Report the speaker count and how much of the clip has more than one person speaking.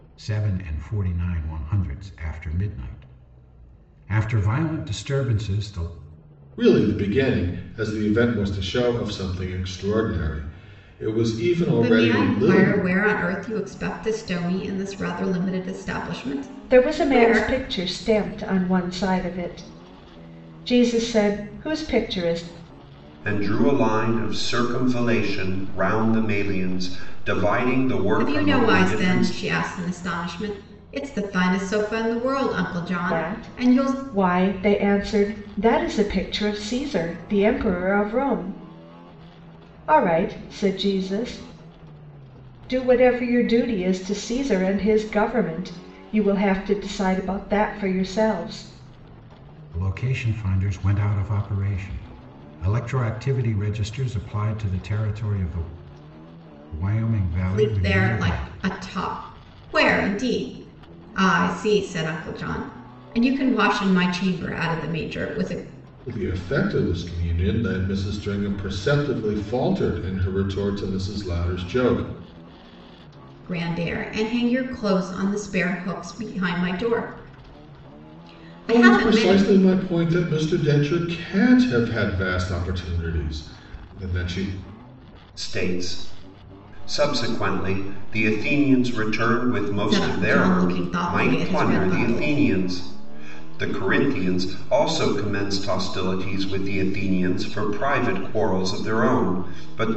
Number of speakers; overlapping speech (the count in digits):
5, about 8%